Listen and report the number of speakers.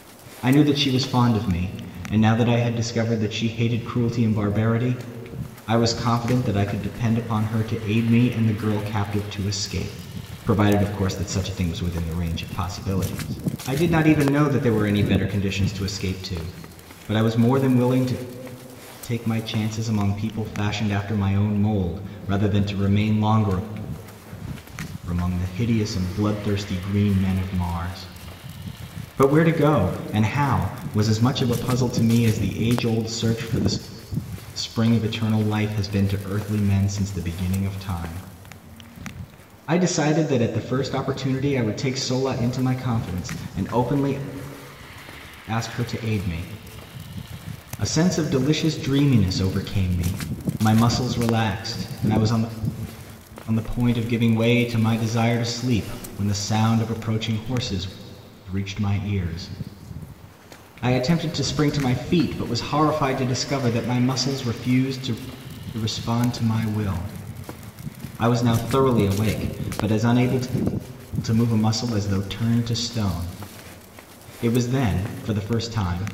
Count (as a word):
one